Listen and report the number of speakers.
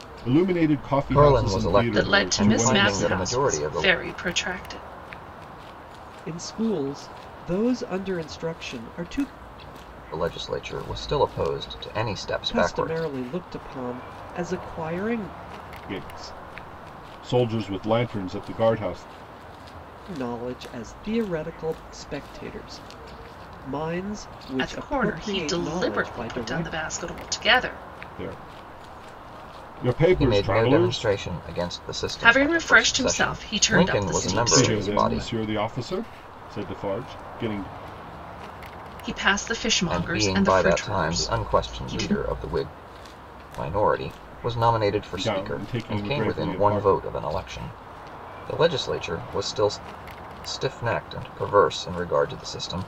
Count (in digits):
4